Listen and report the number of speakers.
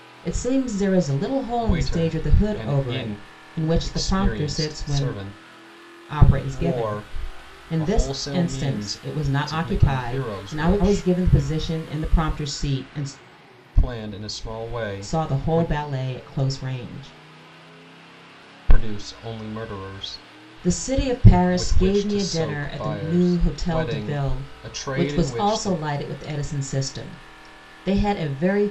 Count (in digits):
2